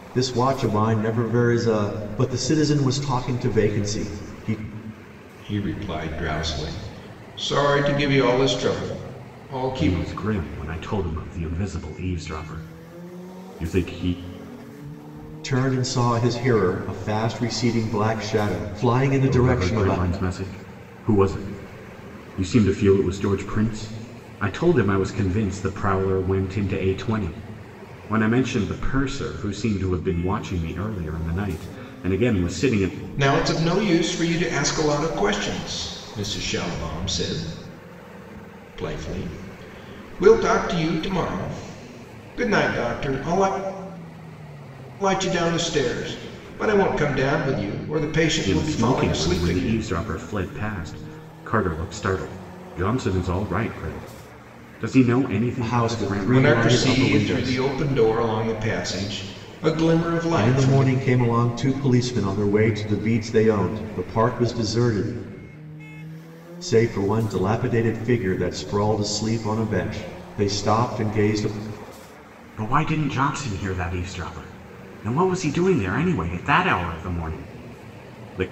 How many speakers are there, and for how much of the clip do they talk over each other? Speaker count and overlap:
3, about 7%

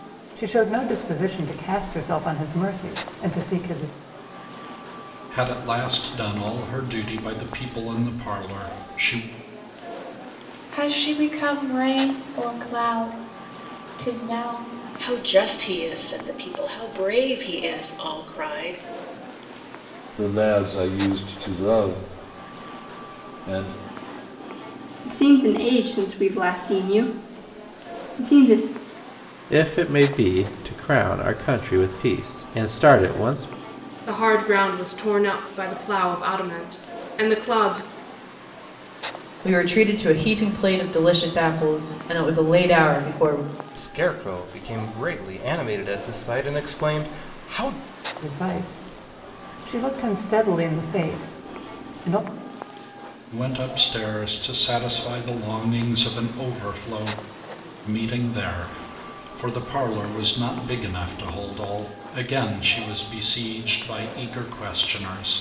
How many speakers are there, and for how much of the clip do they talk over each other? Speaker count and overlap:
10, no overlap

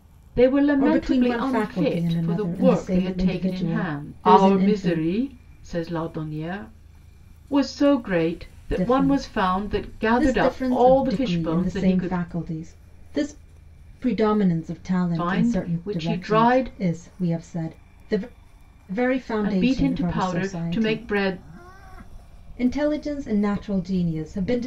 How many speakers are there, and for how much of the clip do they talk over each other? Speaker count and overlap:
2, about 46%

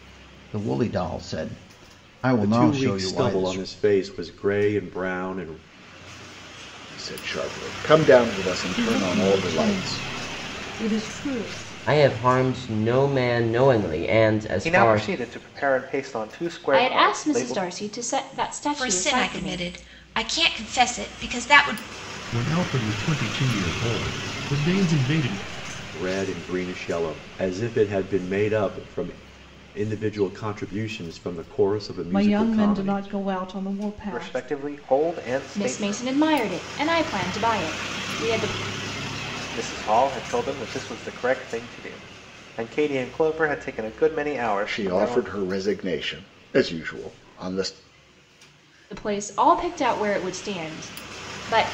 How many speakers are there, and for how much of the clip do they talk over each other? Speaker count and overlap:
9, about 15%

